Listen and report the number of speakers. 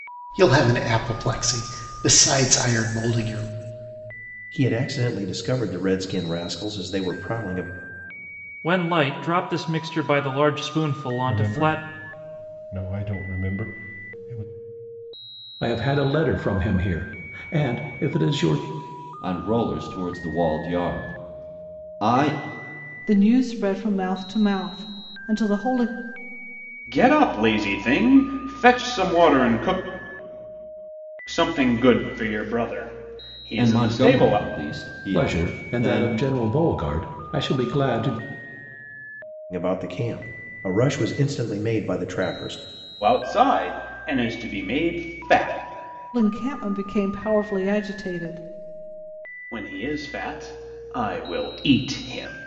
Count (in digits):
8